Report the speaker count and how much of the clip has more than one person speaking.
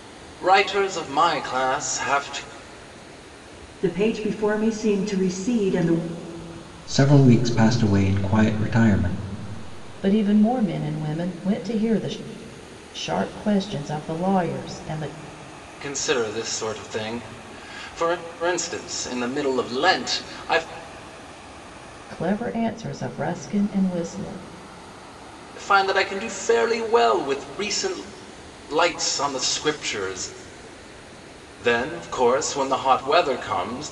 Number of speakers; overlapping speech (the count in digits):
4, no overlap